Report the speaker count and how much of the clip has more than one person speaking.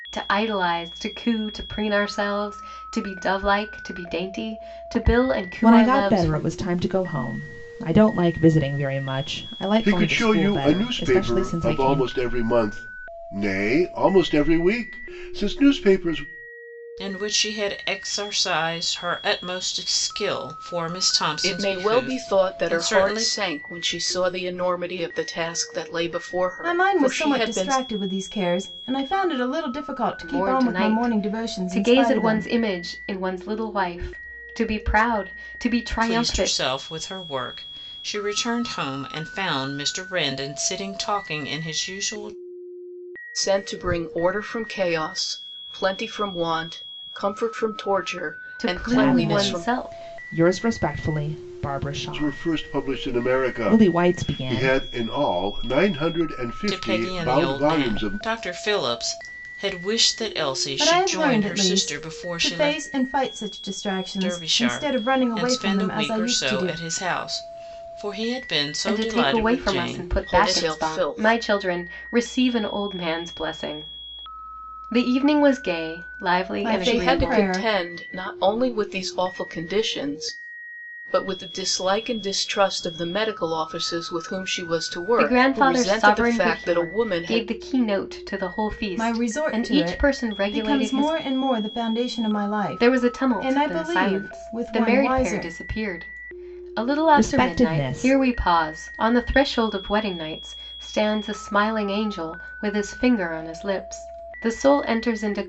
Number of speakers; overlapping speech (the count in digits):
6, about 30%